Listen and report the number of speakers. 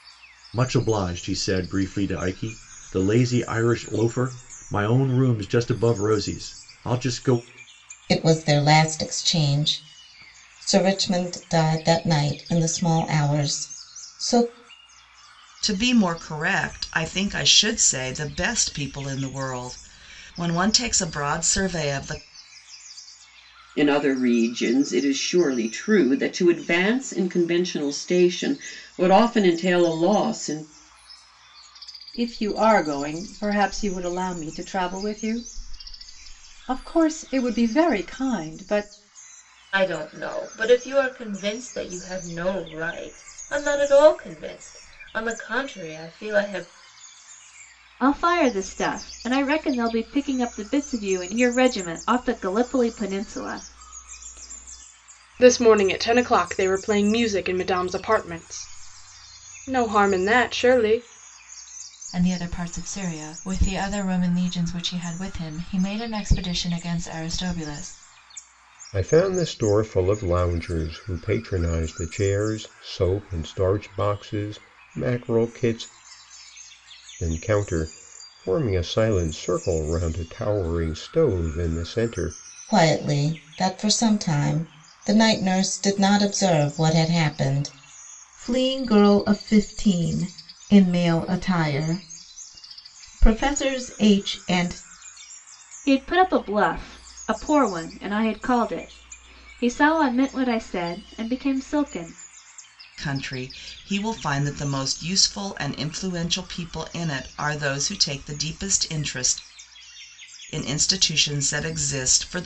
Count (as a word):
ten